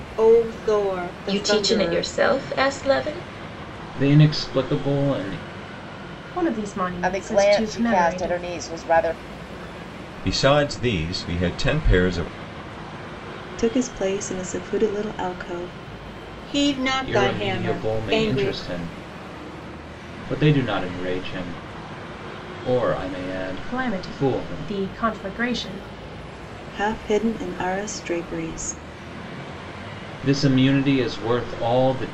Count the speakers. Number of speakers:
7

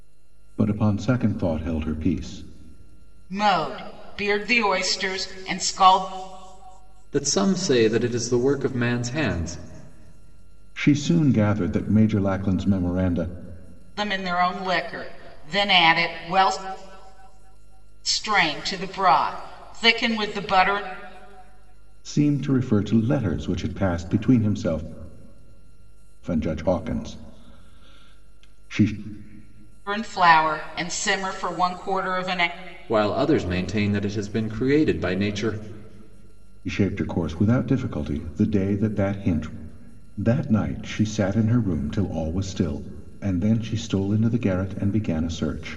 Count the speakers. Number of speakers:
3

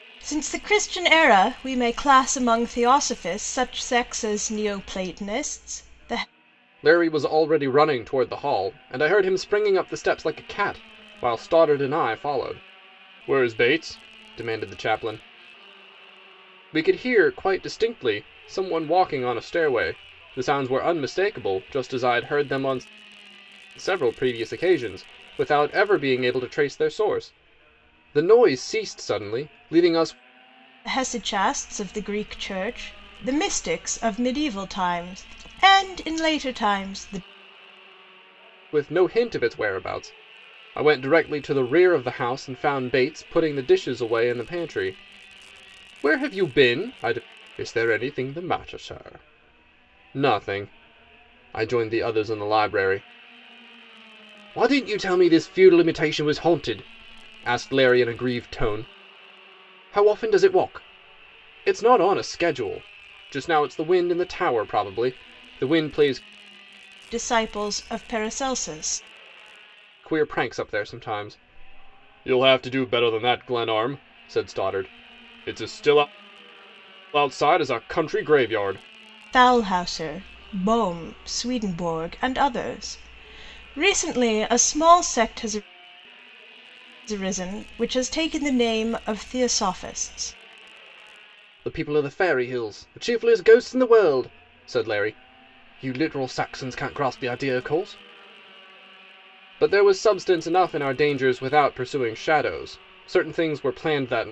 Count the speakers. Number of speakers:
2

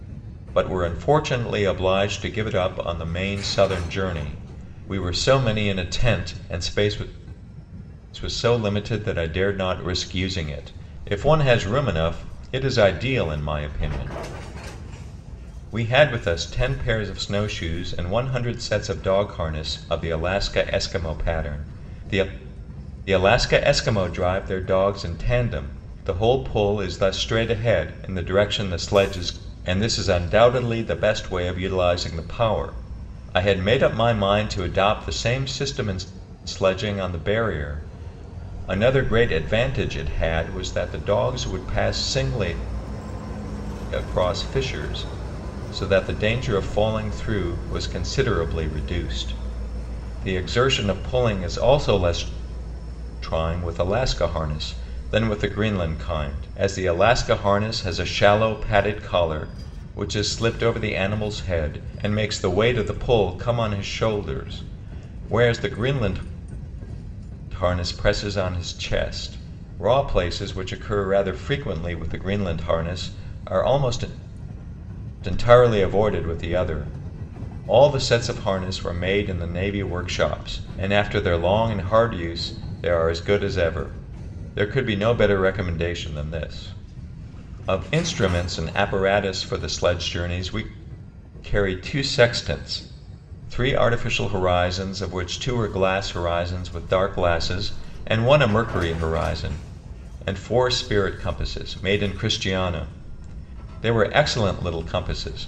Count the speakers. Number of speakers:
1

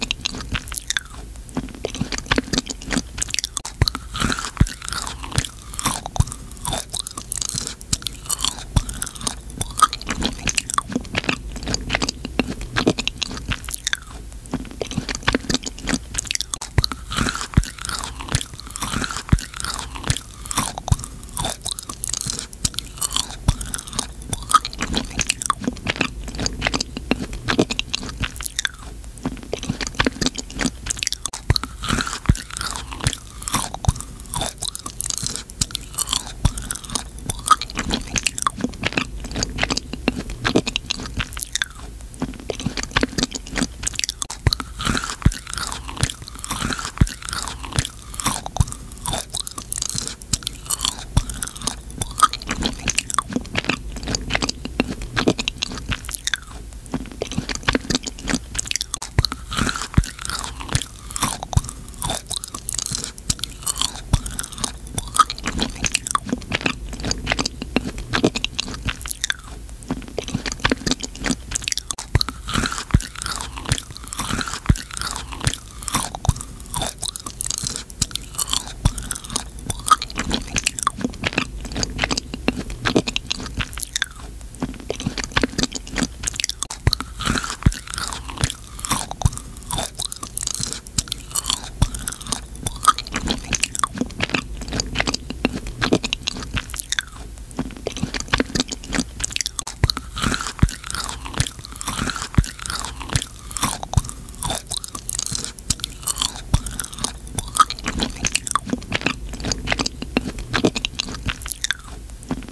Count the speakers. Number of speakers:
0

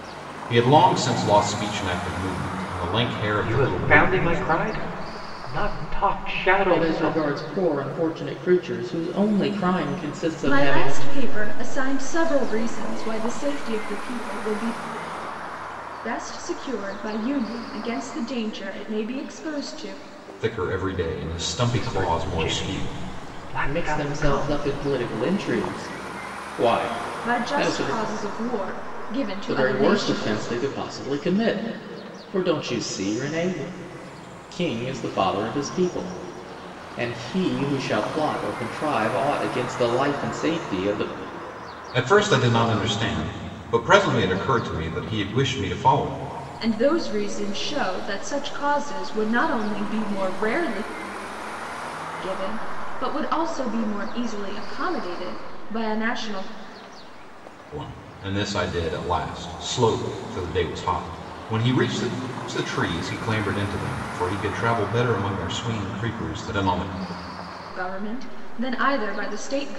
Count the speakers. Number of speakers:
4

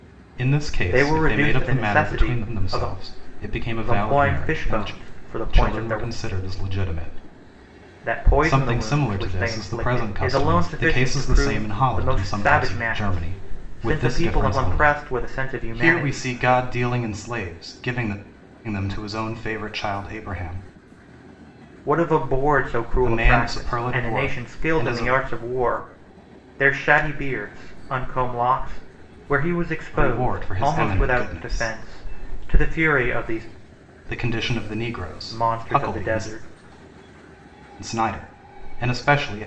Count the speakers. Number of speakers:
2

